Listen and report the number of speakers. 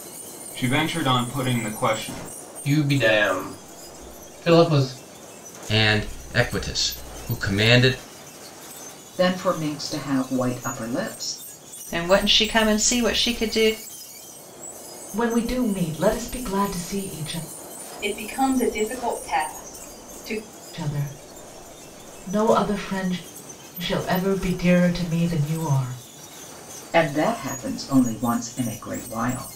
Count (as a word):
seven